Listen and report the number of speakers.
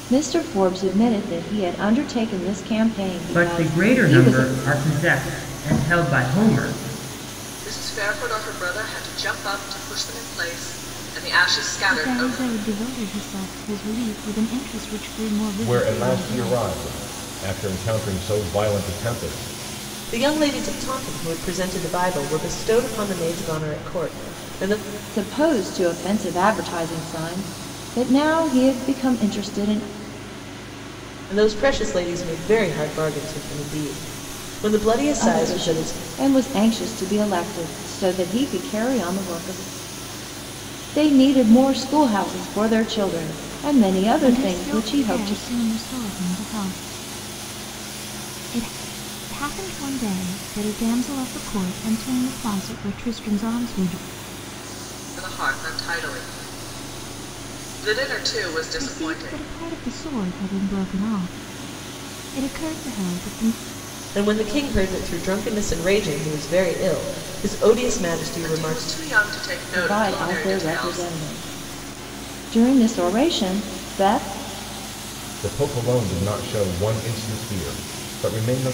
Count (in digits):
6